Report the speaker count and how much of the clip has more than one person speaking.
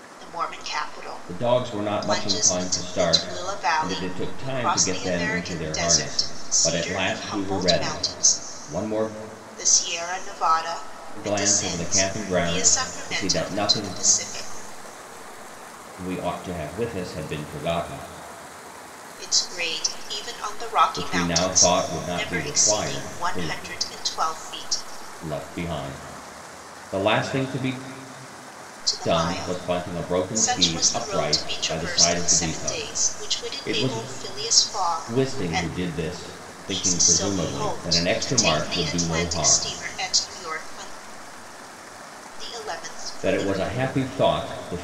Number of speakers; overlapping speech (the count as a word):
two, about 46%